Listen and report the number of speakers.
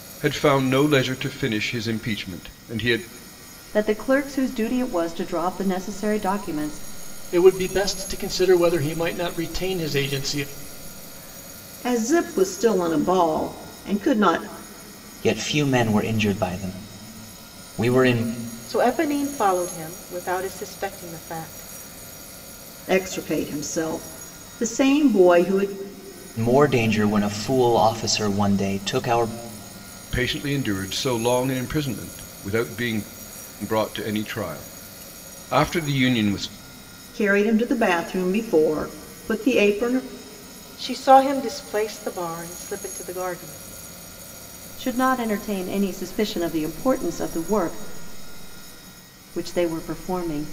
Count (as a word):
six